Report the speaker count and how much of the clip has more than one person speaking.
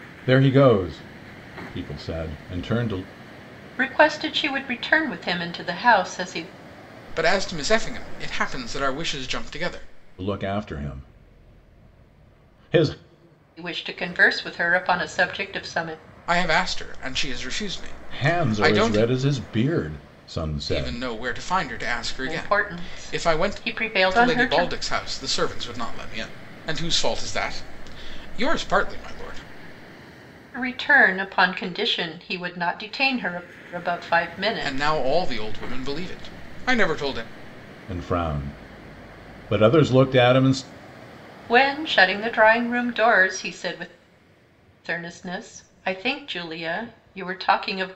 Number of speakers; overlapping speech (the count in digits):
3, about 8%